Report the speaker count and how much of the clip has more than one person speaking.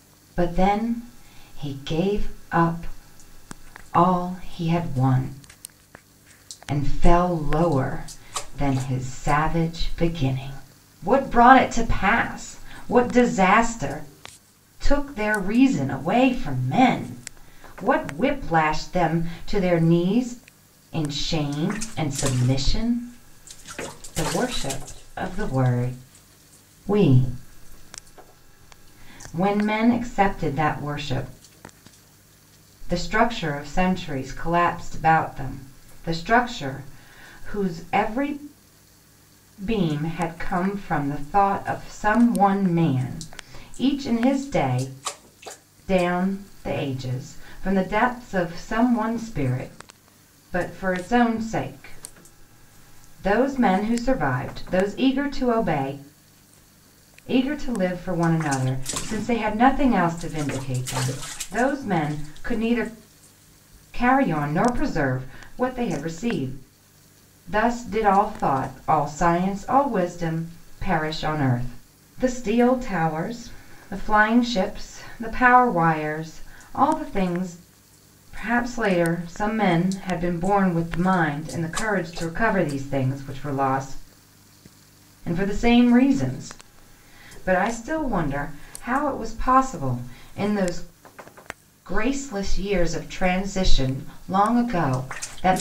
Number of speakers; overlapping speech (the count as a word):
one, no overlap